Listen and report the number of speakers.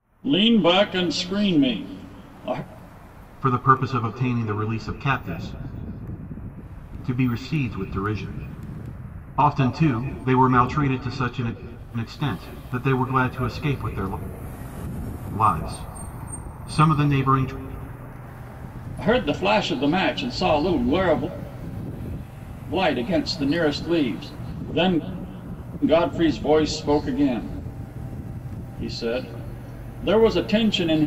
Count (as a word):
two